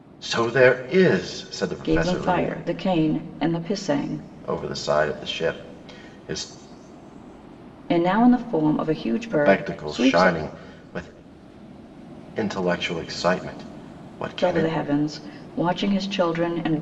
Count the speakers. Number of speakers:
two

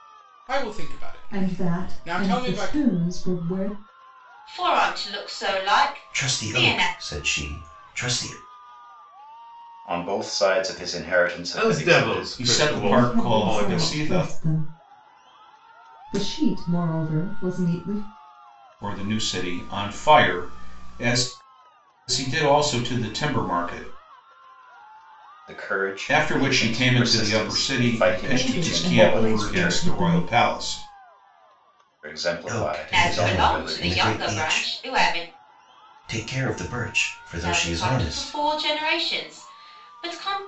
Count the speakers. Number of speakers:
seven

